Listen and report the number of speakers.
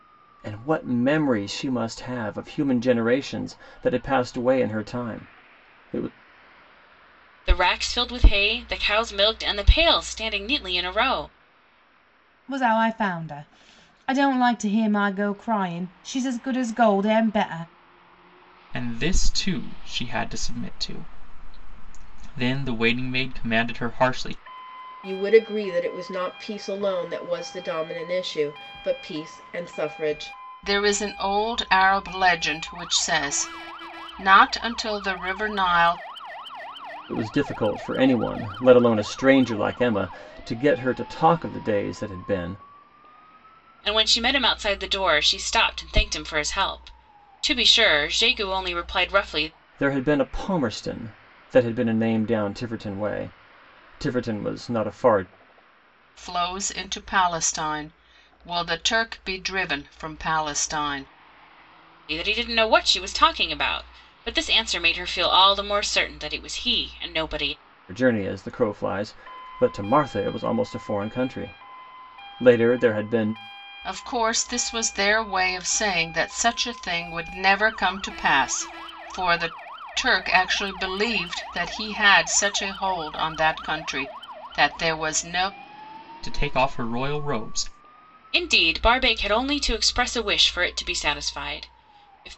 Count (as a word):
six